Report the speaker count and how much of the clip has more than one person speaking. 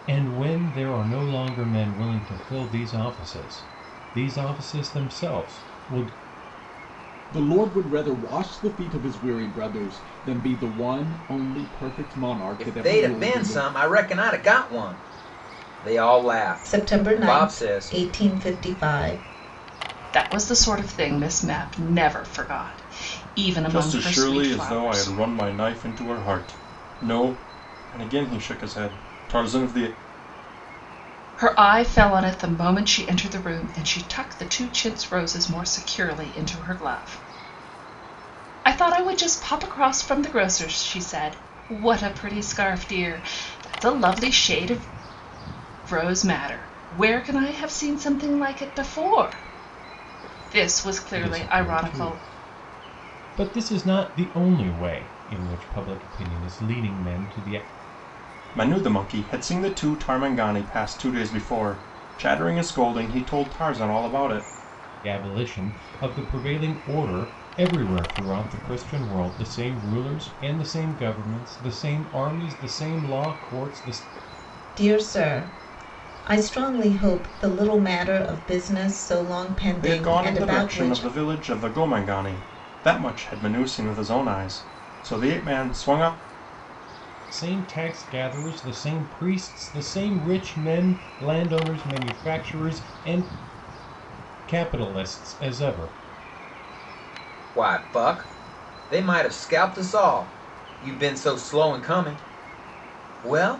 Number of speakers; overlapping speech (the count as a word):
six, about 6%